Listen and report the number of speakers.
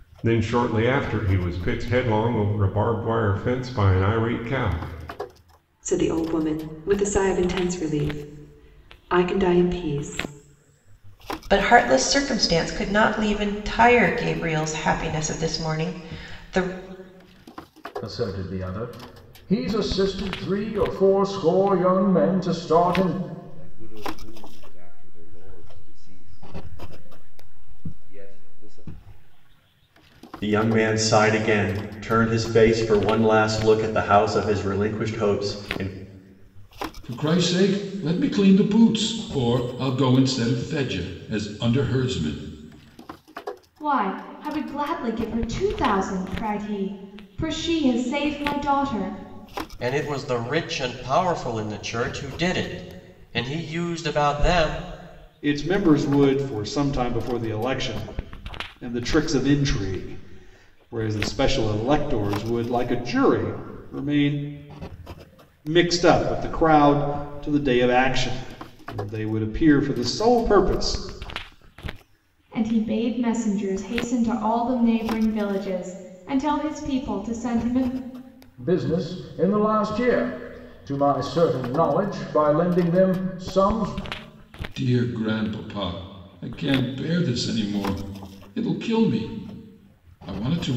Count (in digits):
10